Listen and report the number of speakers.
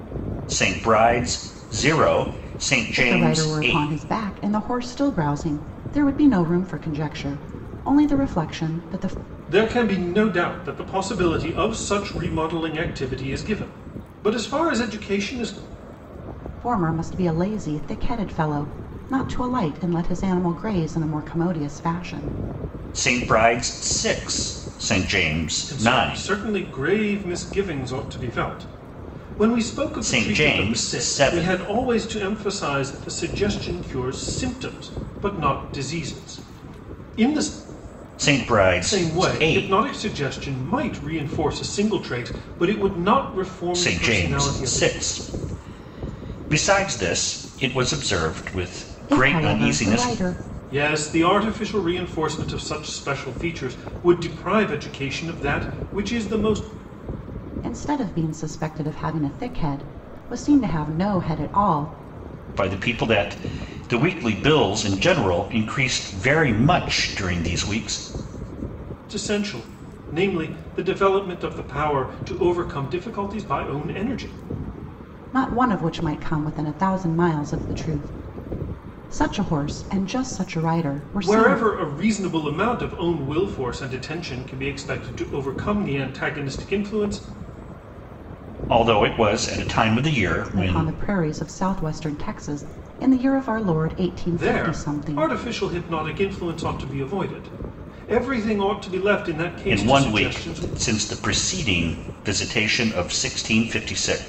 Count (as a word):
three